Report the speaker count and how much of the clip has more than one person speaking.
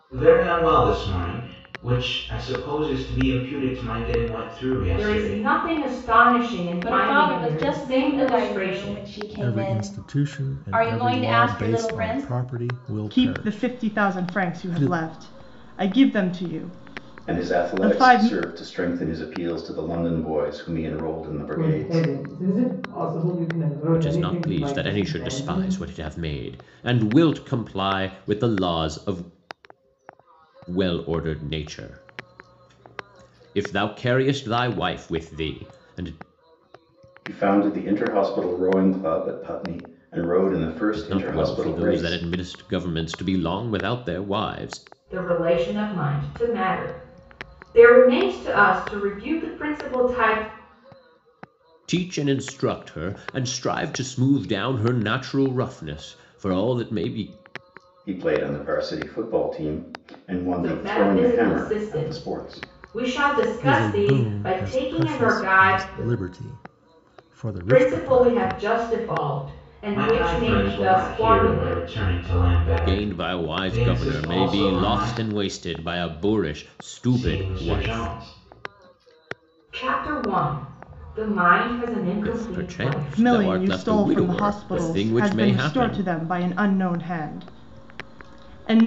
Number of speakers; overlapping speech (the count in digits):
8, about 31%